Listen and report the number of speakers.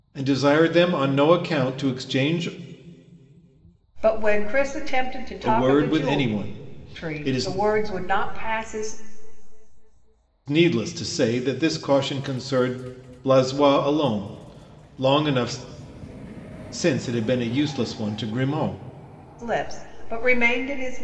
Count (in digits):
2